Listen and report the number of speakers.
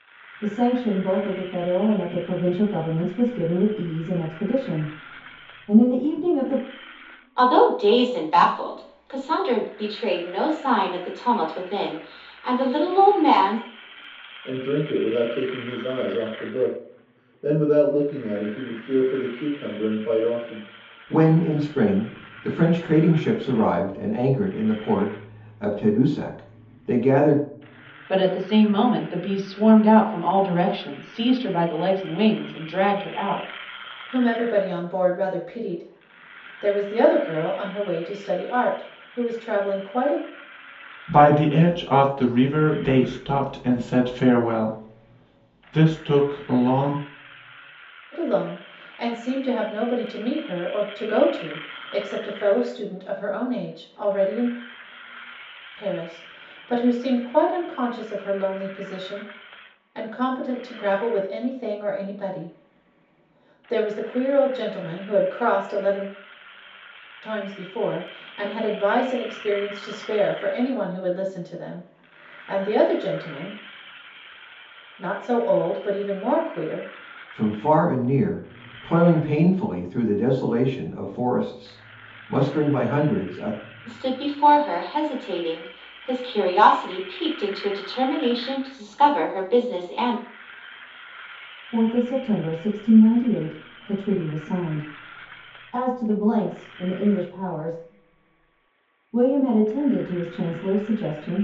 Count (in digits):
7